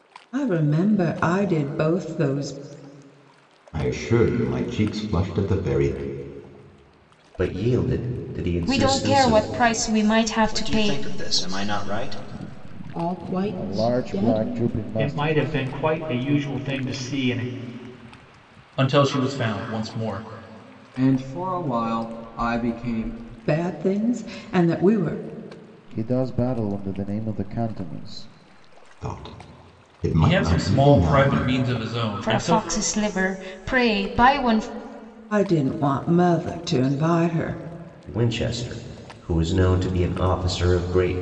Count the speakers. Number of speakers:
10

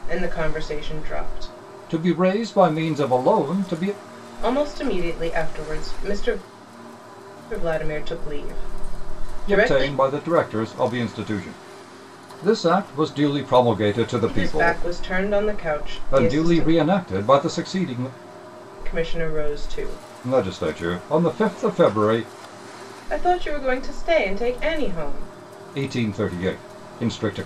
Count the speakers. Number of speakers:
2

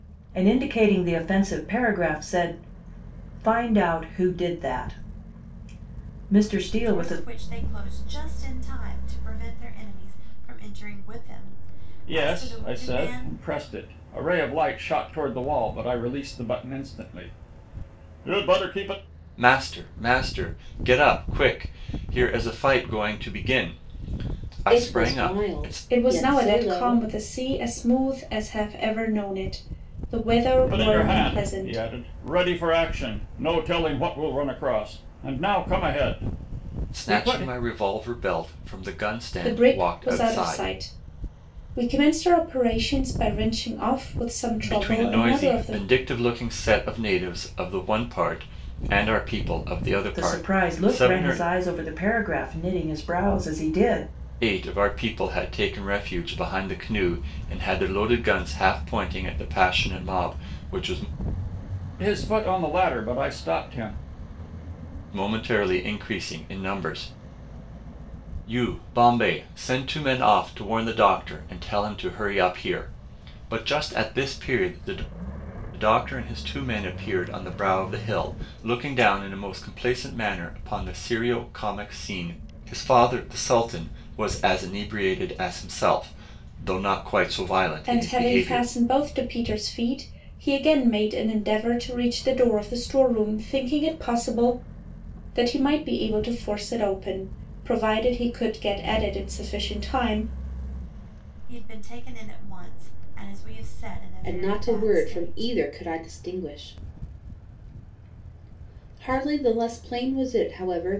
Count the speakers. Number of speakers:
6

